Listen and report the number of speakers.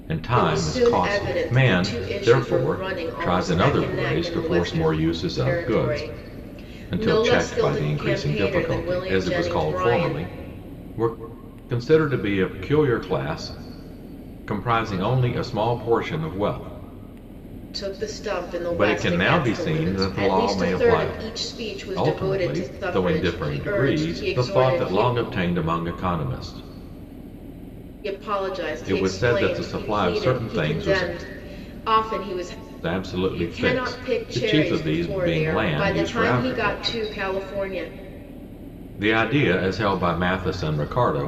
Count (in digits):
2